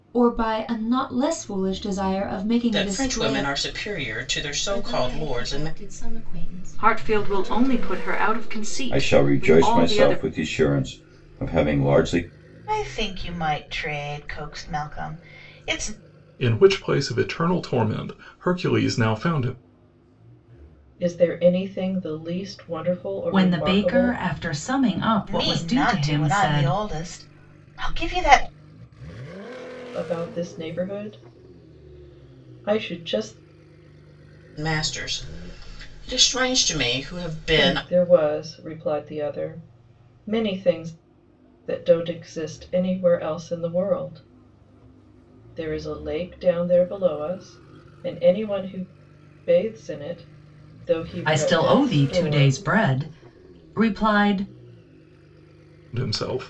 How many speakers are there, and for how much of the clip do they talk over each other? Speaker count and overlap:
nine, about 15%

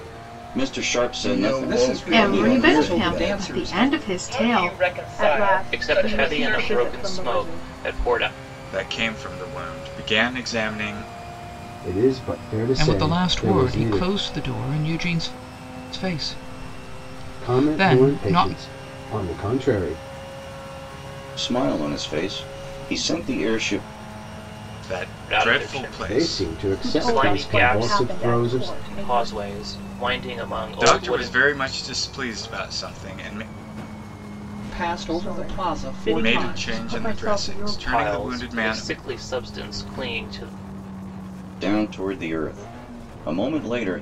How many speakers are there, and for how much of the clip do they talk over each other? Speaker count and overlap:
ten, about 39%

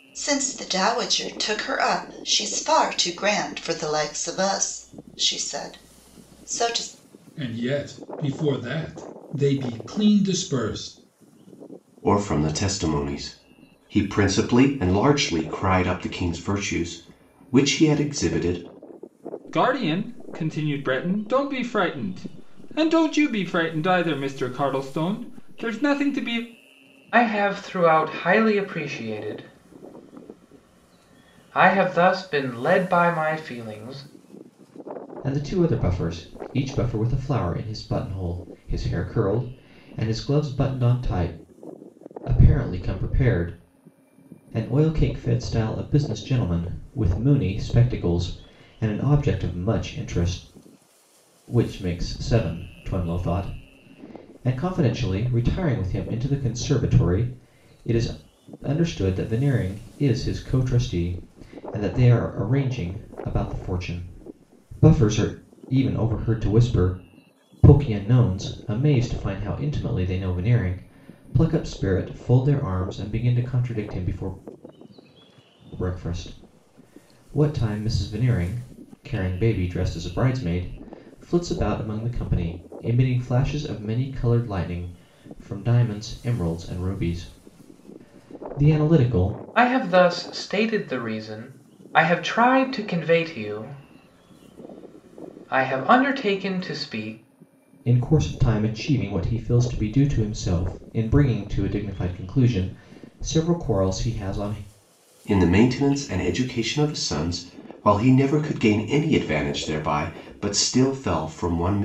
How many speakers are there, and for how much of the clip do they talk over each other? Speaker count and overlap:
six, no overlap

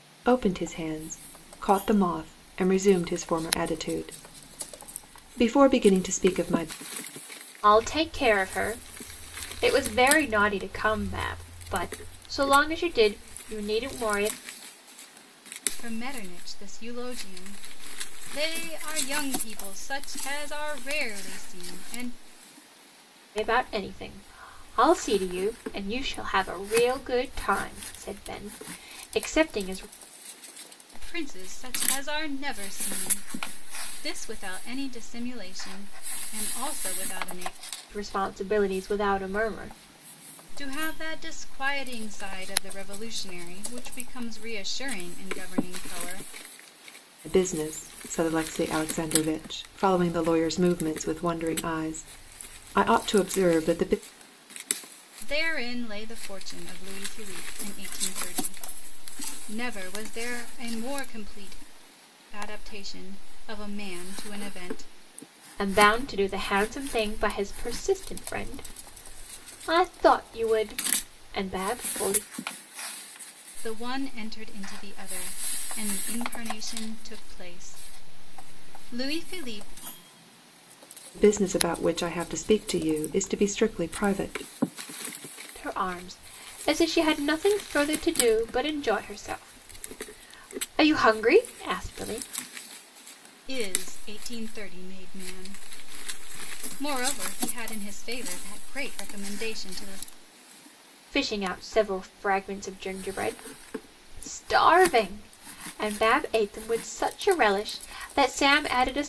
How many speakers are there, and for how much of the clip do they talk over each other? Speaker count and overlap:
three, no overlap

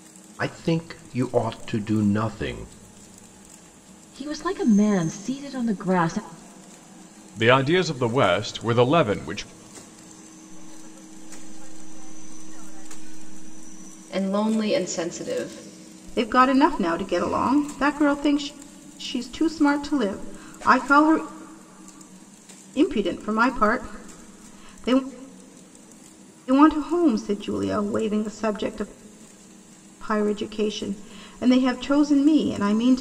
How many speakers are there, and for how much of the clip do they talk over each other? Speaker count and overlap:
six, no overlap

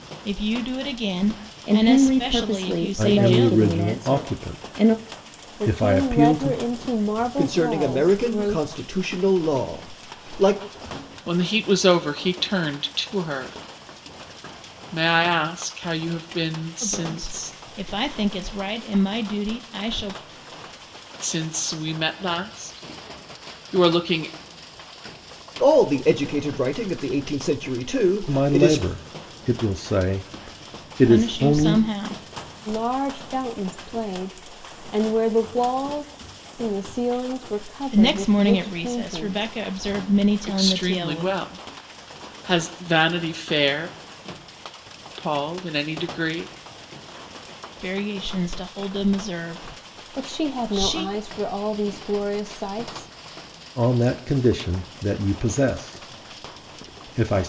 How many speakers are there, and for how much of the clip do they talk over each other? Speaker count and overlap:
six, about 20%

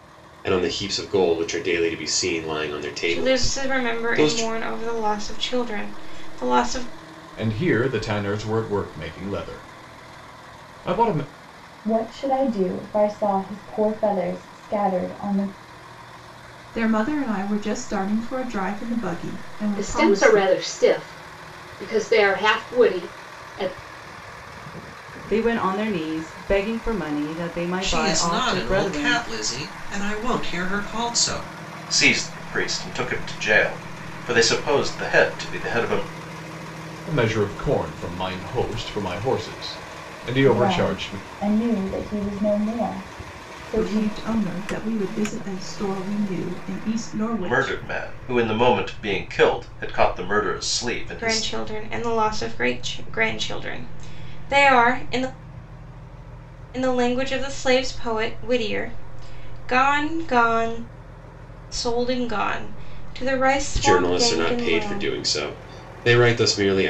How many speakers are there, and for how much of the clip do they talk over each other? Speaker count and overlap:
nine, about 10%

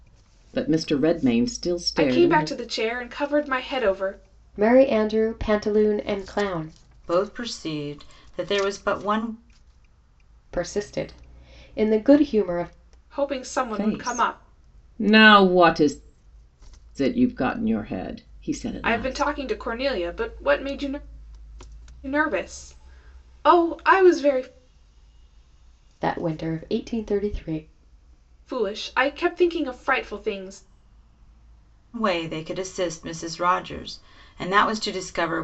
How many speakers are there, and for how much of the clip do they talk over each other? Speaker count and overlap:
four, about 5%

